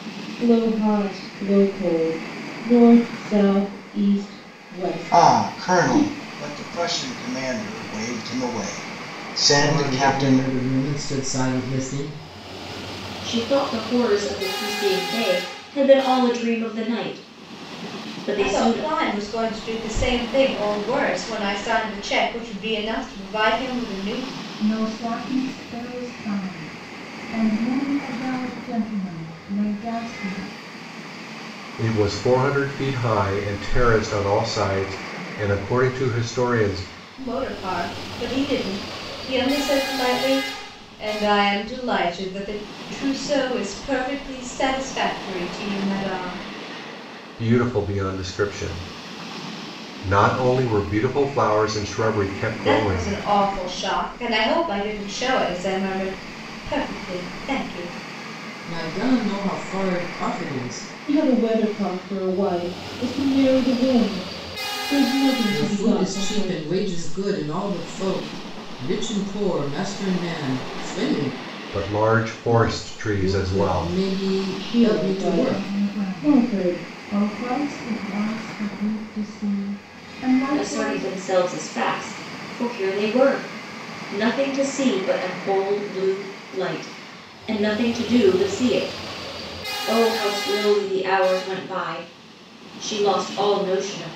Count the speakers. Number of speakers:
7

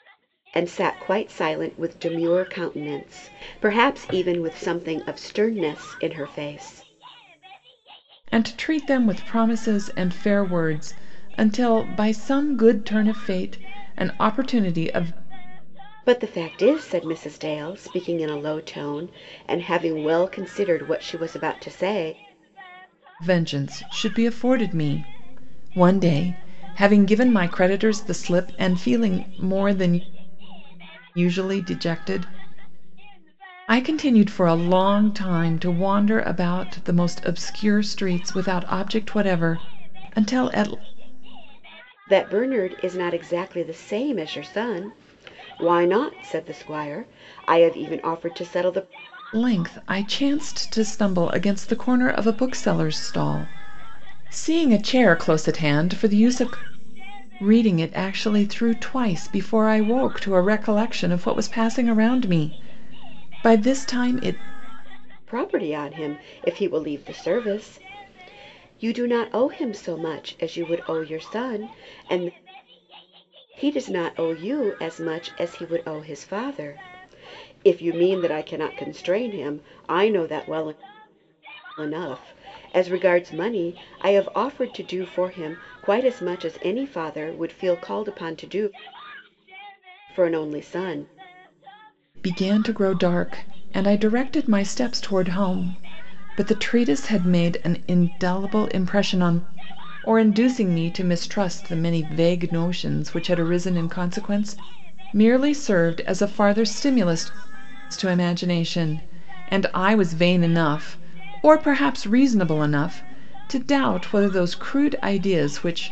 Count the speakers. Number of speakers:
2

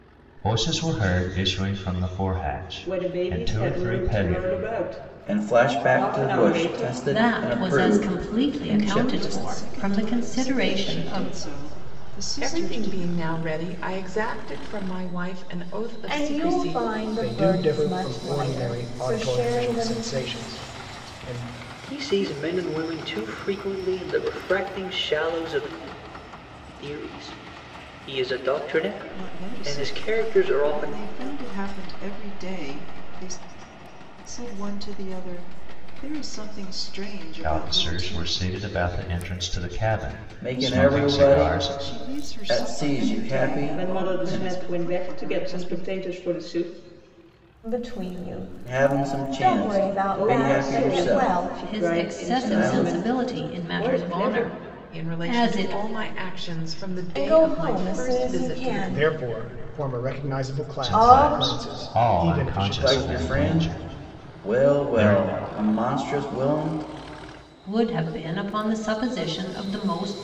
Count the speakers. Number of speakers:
9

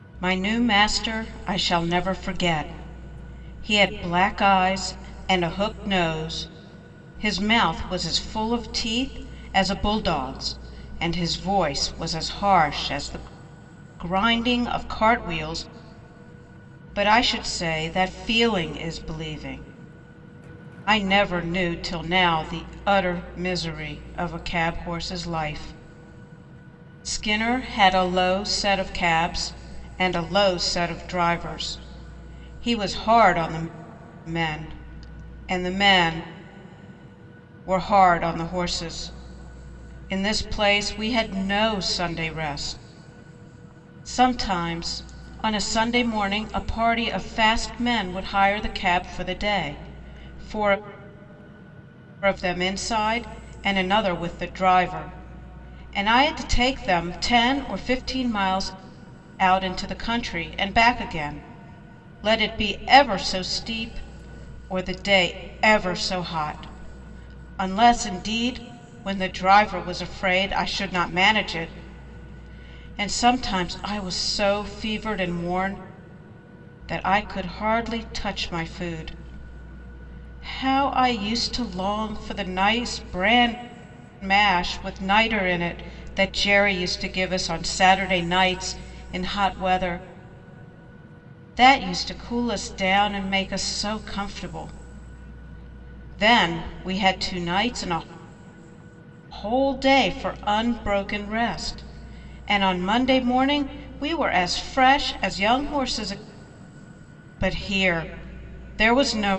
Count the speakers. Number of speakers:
1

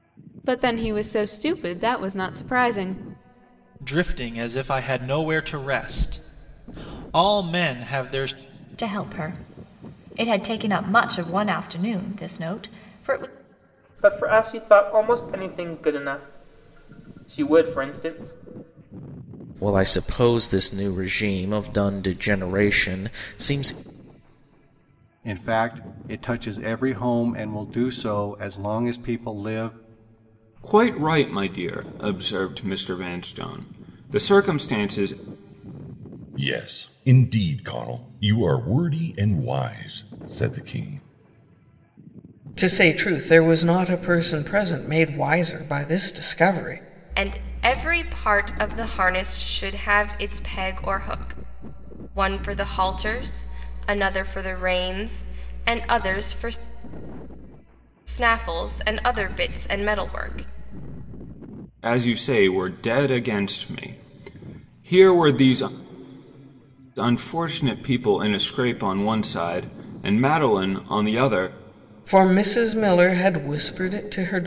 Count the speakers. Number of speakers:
10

